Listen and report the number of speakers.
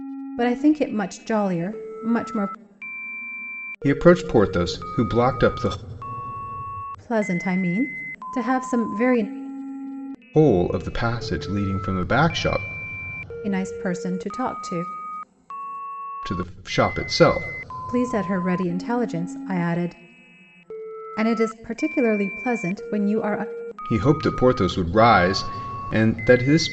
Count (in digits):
2